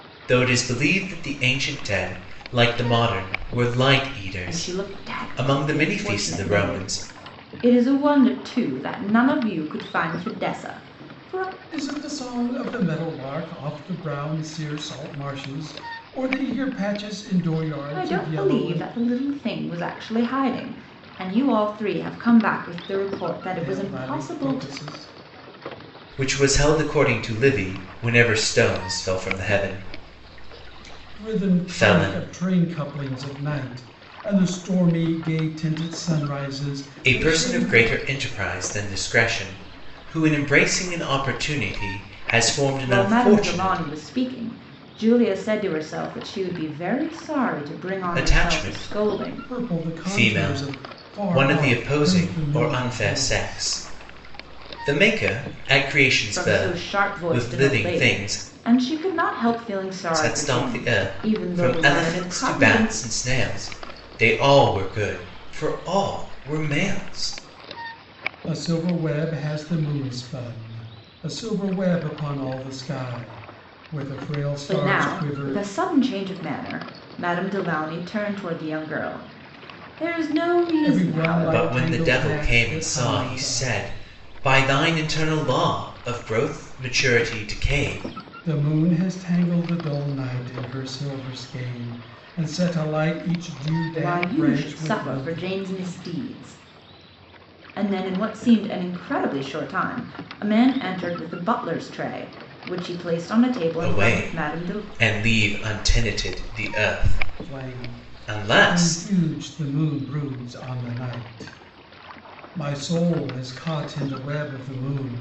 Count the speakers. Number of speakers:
3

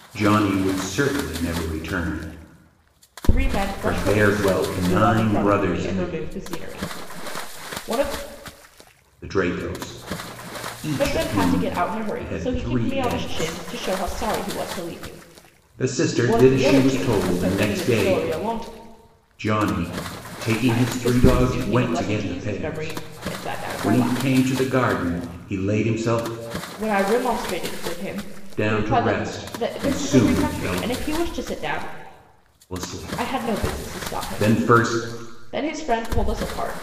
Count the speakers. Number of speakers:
2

